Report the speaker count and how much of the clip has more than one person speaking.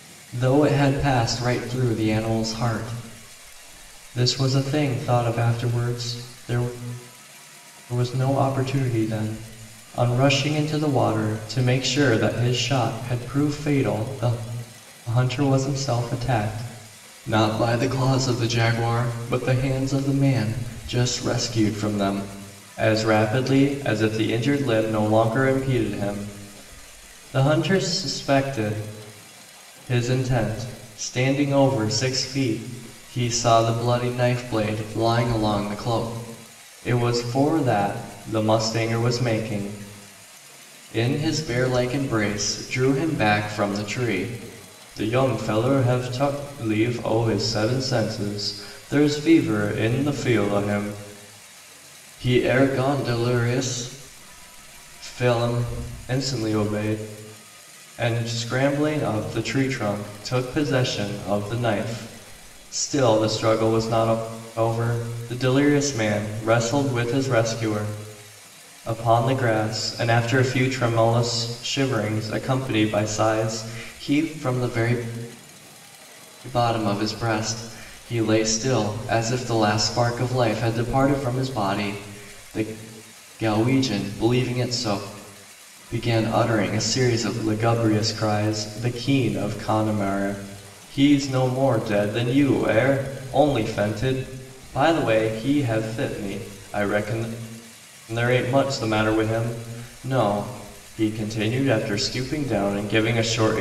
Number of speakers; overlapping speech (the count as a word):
one, no overlap